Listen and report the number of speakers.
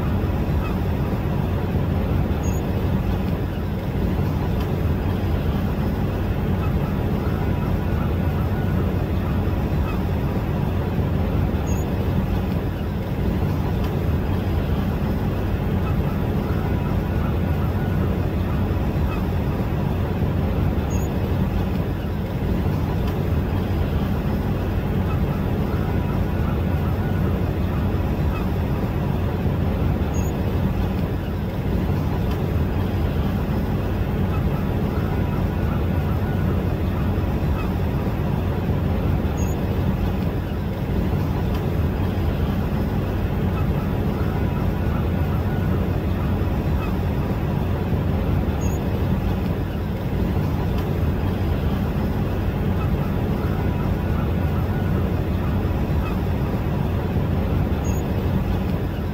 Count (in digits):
0